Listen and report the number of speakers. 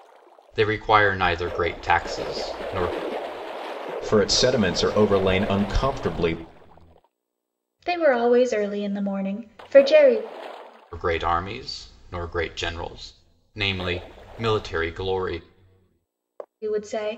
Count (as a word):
three